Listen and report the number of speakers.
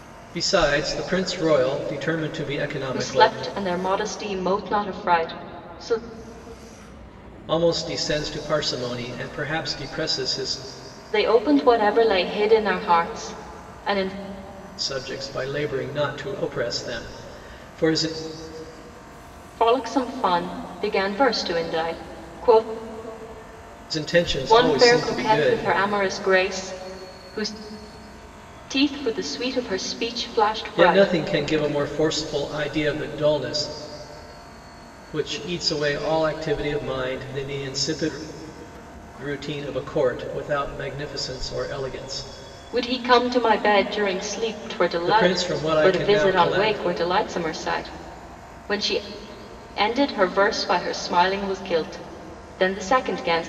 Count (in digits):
2